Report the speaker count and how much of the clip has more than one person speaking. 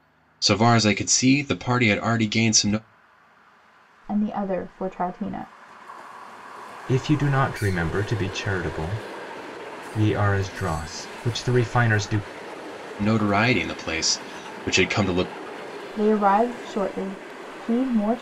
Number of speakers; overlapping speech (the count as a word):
three, no overlap